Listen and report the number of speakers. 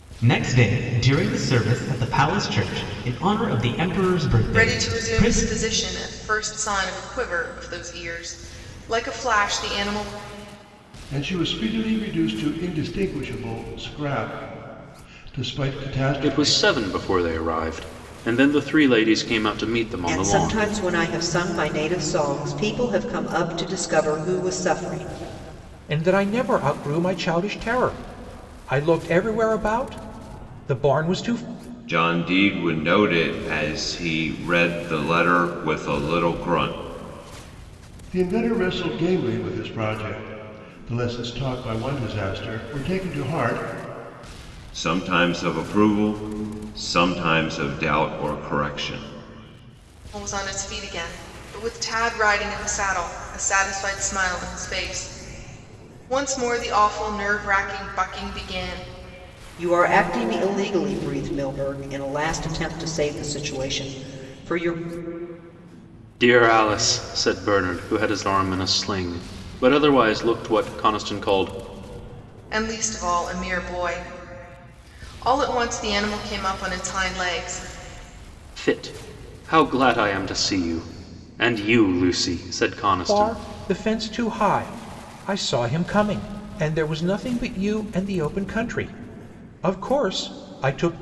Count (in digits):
7